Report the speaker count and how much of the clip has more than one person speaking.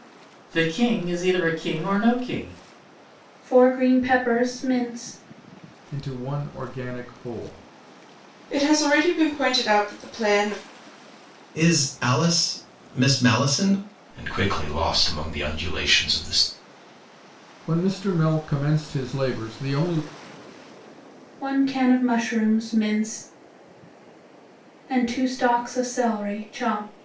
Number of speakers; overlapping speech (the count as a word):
six, no overlap